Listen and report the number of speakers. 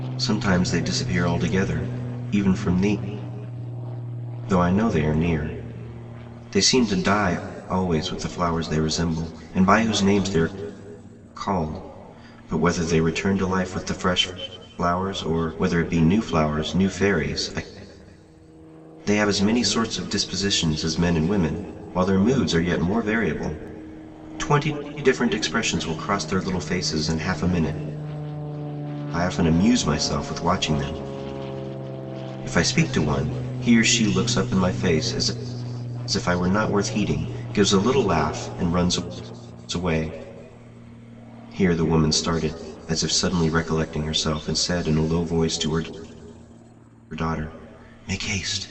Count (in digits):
1